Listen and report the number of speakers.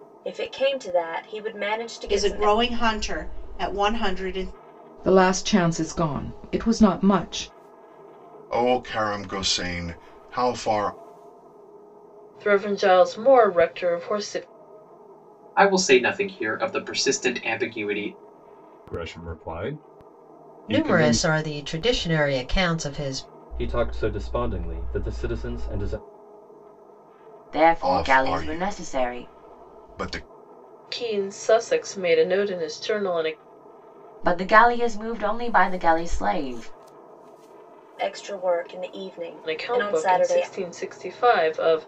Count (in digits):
10